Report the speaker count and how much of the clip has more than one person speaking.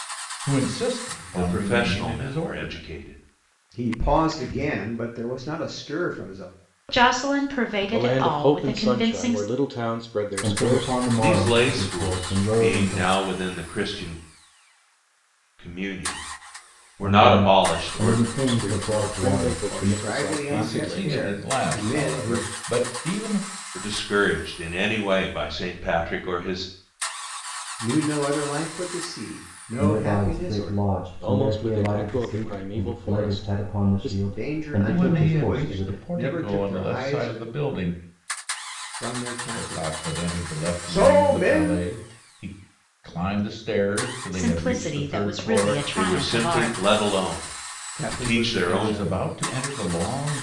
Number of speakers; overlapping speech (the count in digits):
6, about 48%